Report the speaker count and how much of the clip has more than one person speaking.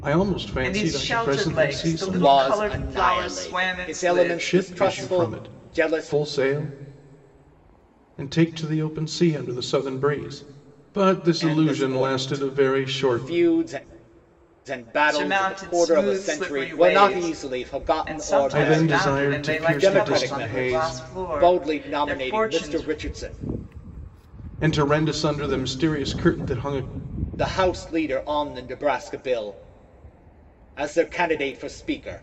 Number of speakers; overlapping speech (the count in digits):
3, about 46%